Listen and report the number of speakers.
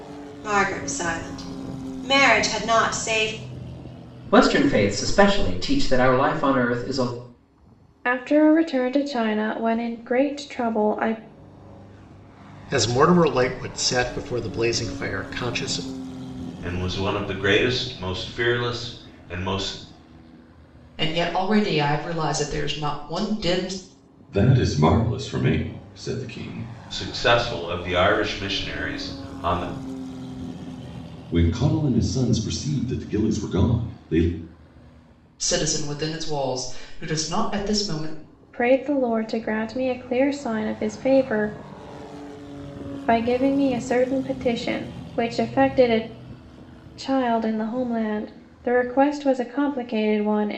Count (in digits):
7